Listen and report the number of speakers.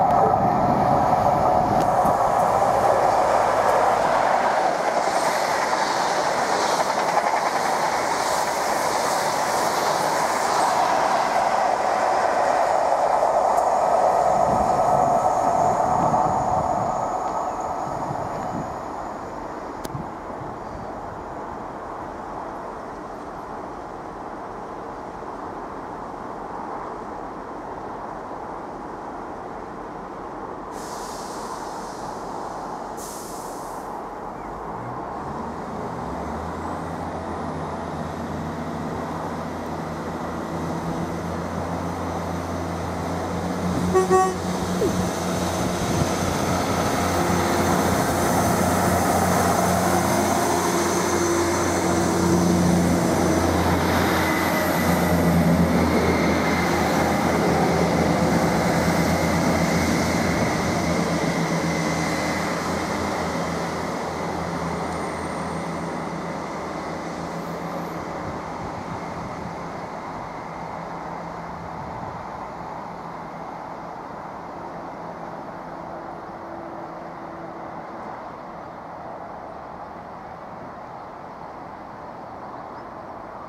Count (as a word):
zero